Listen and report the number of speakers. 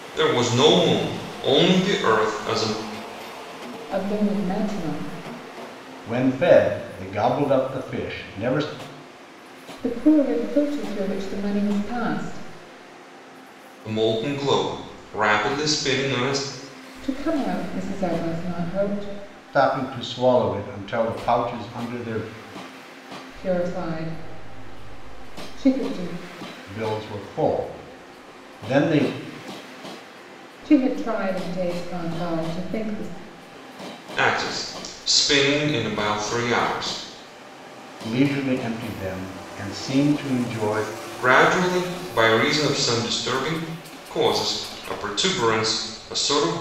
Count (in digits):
3